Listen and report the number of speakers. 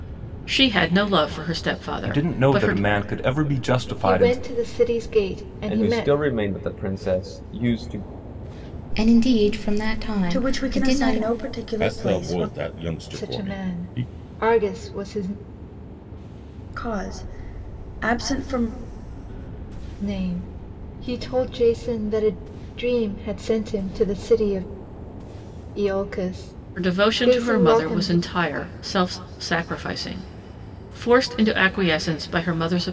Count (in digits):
7